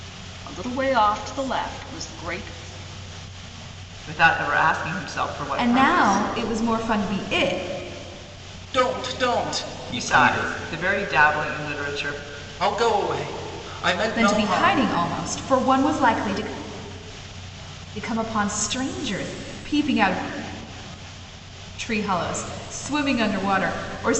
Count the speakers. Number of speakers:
4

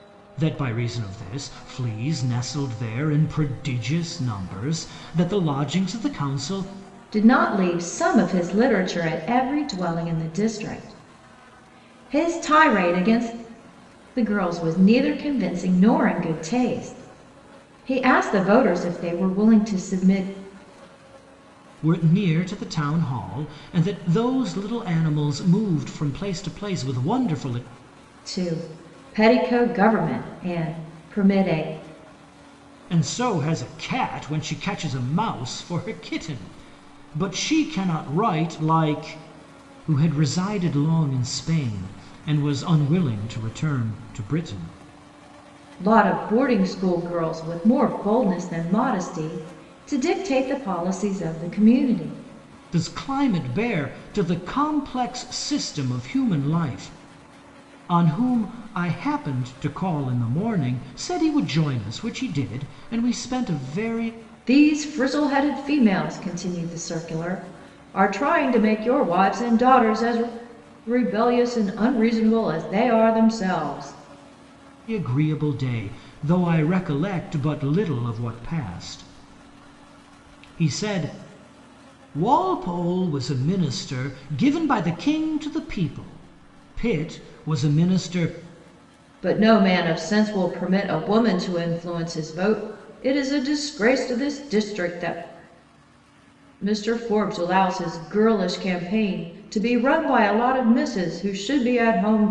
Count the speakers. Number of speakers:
2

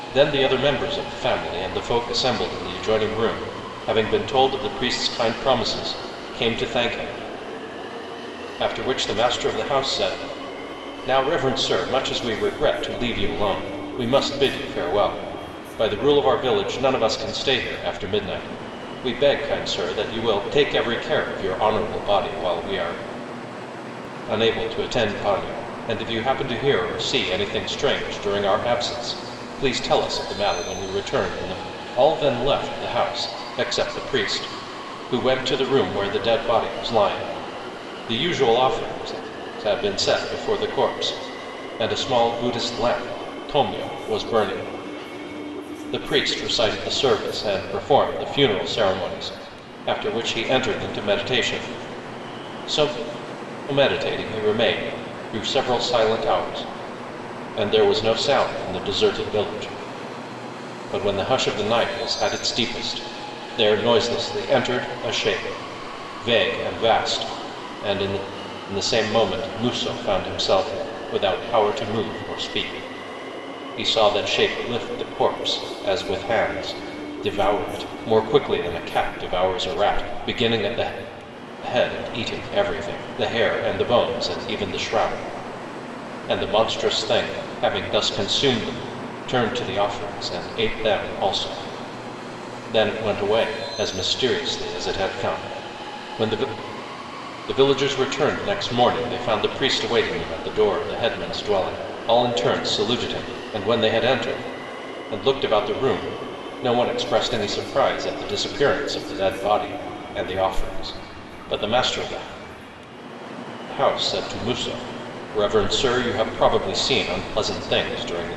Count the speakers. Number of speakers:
1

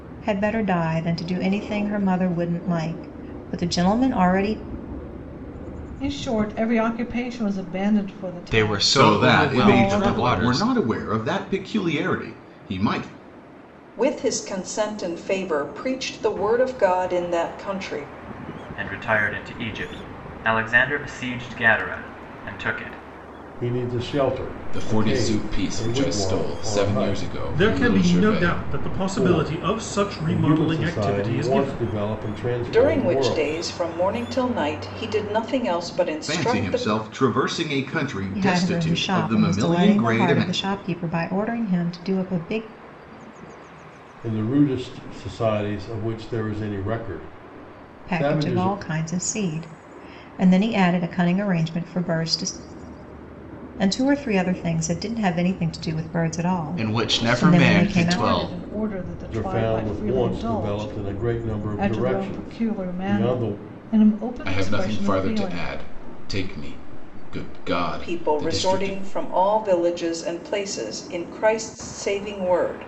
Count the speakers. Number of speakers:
9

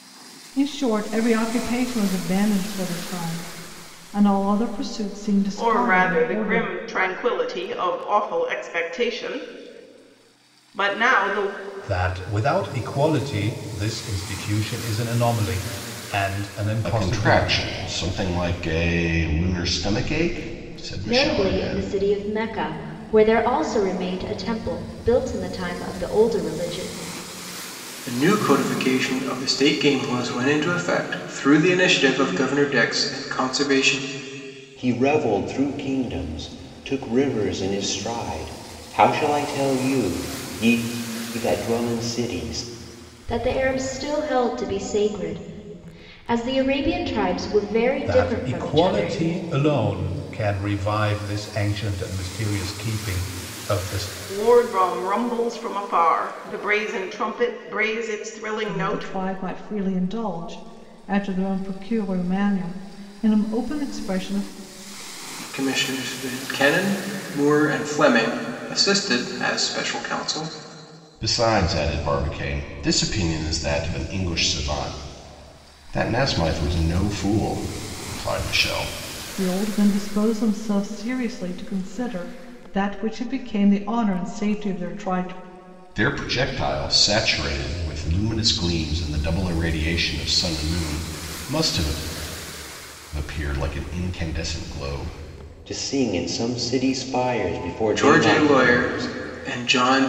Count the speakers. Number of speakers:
7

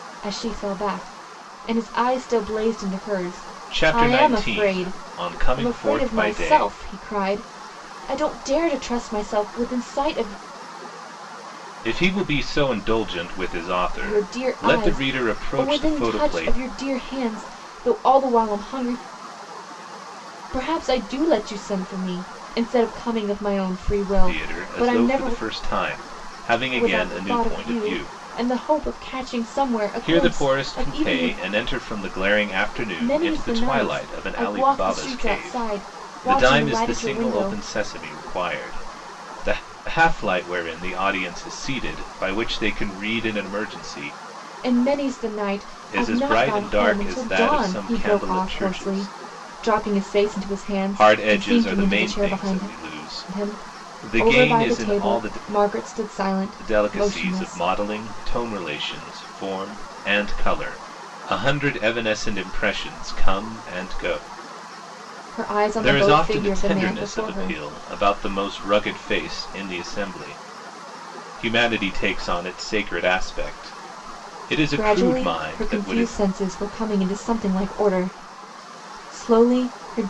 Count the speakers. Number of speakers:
2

